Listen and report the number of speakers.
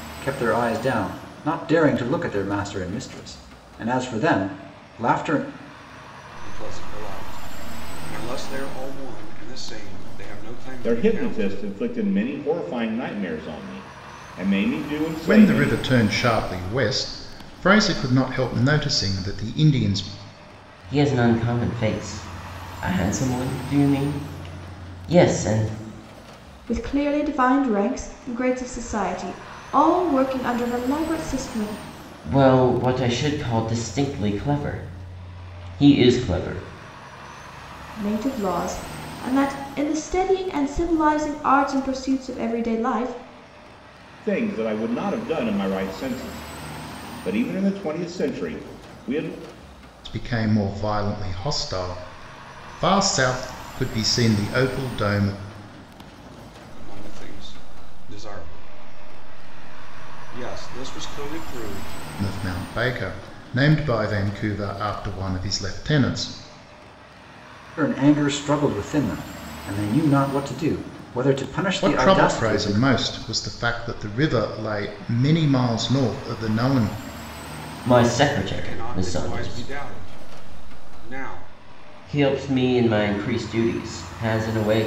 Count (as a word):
six